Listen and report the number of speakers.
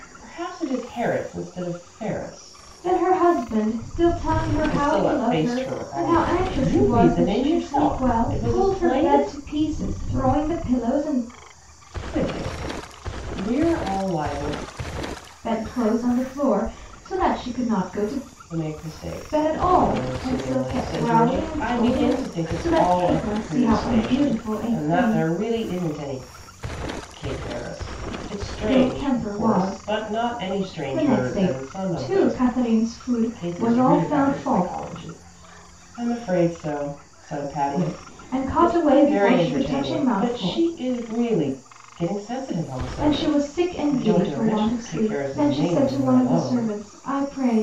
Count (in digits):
2